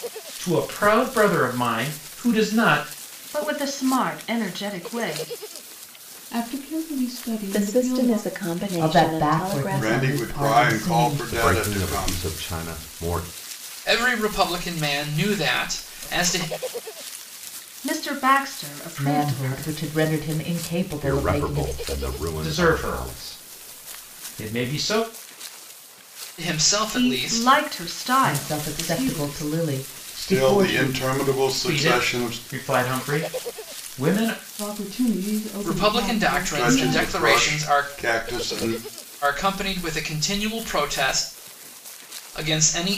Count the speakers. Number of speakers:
eight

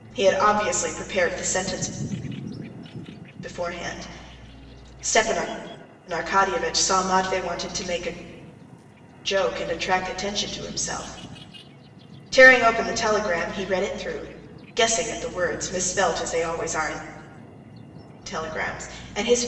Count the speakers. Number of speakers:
one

